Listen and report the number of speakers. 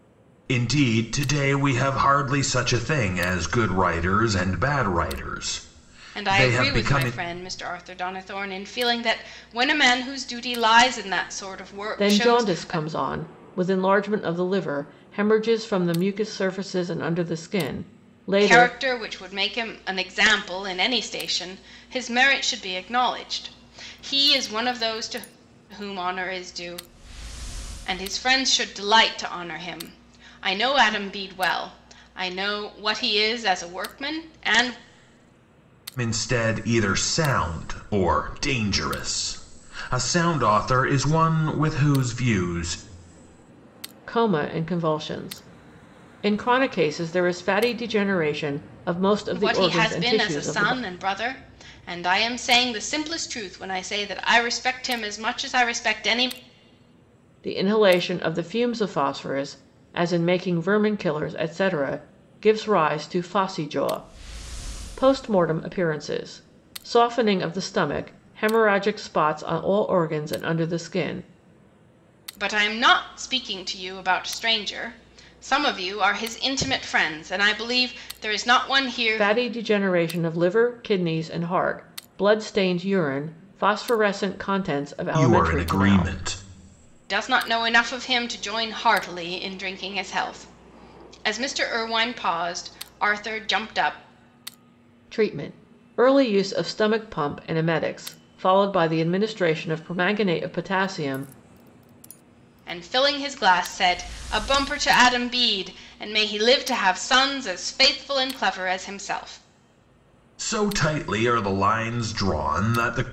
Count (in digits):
3